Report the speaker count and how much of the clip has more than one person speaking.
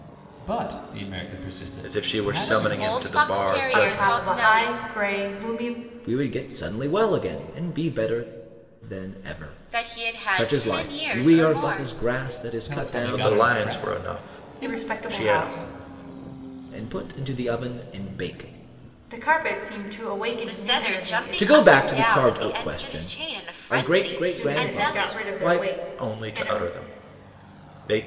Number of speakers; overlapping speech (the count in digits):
5, about 48%